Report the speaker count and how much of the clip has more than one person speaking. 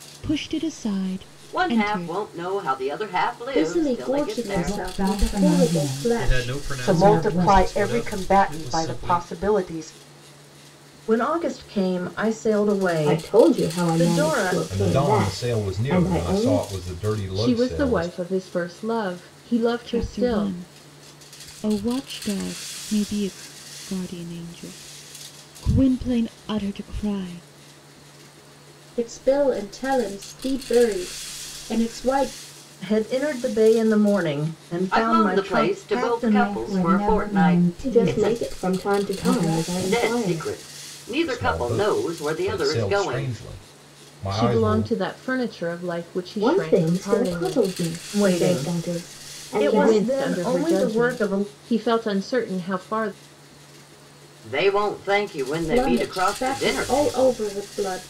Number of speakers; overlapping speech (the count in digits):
10, about 45%